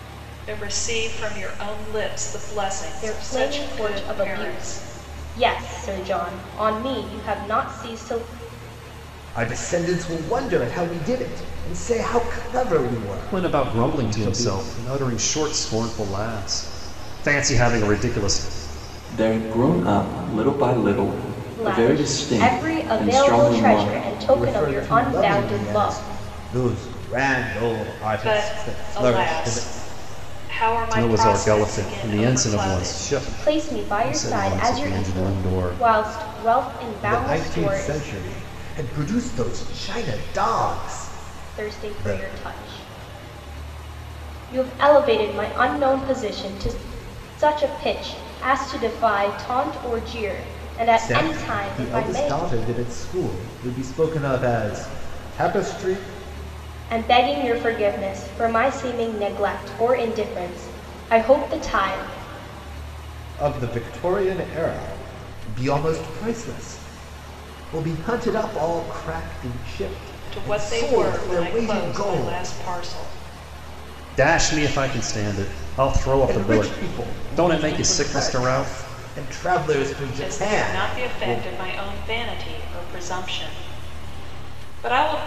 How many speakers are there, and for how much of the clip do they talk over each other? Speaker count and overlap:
five, about 27%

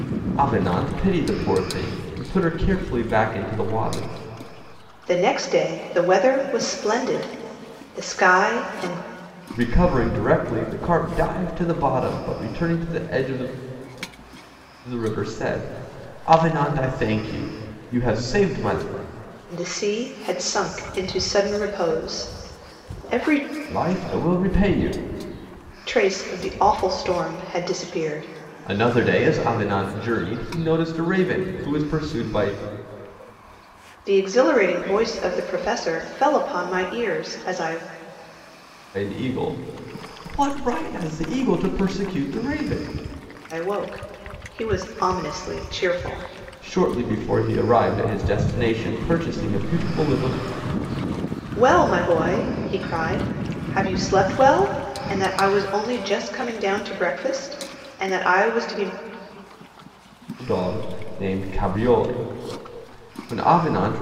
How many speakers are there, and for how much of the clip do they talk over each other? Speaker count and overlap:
two, no overlap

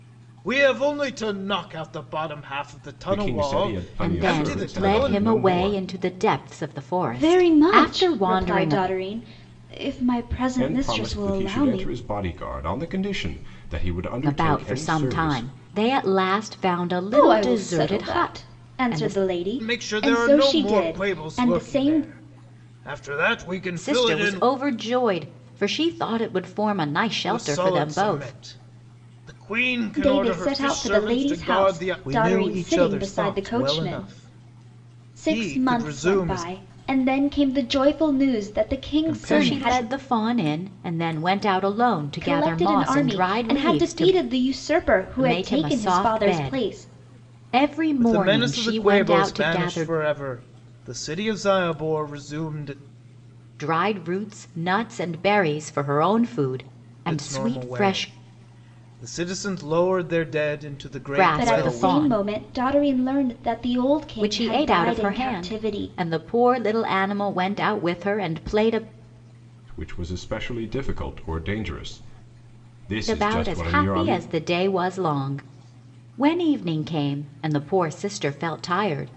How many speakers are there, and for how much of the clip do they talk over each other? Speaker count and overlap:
four, about 39%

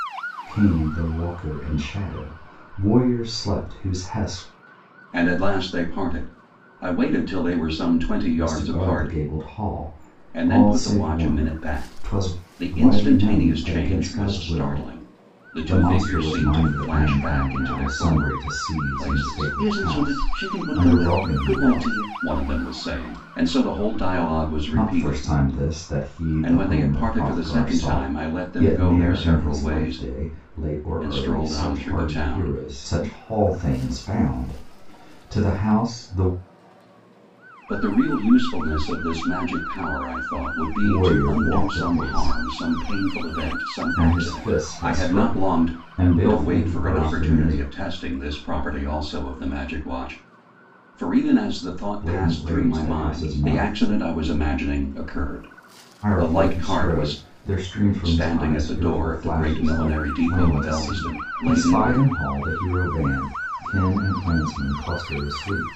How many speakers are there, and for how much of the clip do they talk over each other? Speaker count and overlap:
two, about 43%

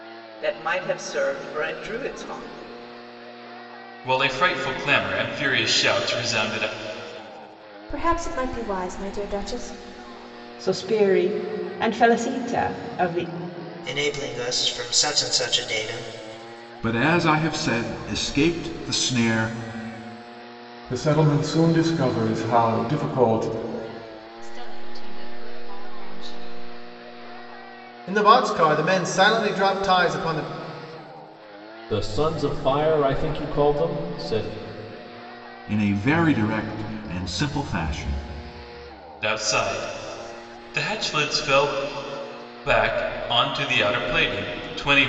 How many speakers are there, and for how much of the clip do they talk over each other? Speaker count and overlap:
ten, no overlap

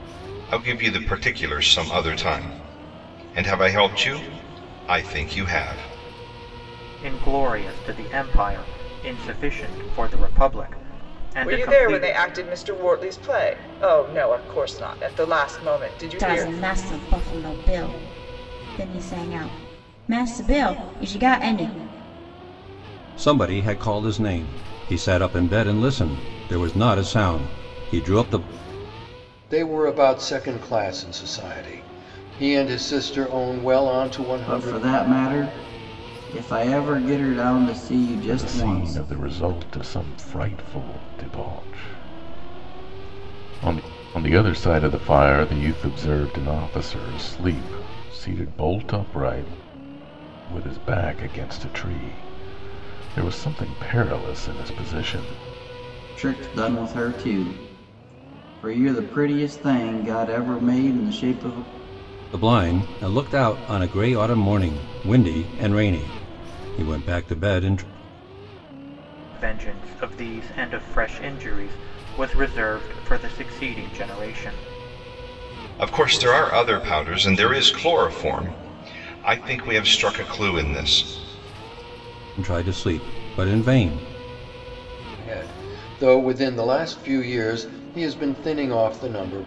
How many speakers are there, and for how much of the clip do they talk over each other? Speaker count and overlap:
eight, about 3%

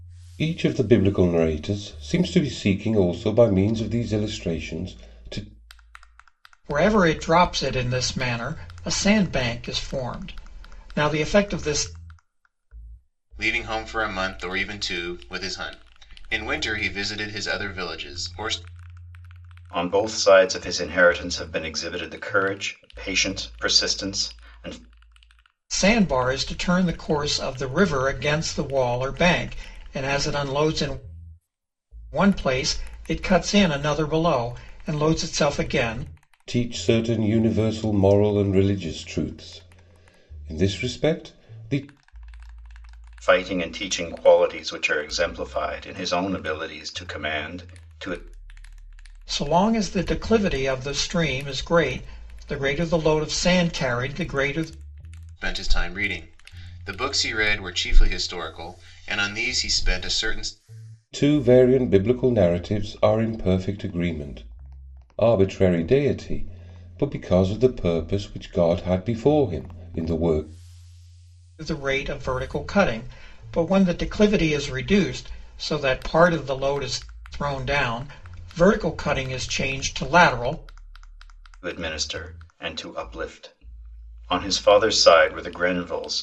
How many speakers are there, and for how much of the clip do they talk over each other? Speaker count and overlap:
four, no overlap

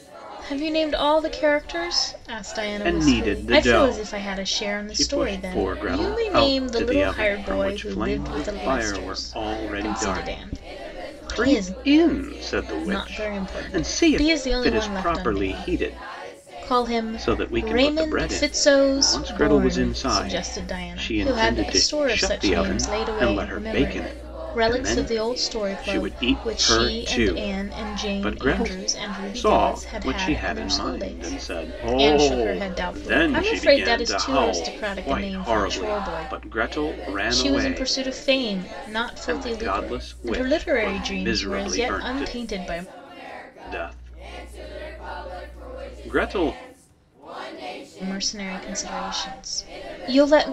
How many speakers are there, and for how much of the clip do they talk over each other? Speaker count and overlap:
two, about 60%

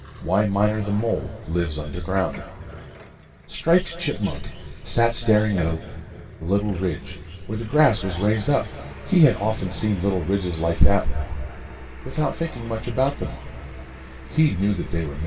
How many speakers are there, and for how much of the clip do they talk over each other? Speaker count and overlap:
one, no overlap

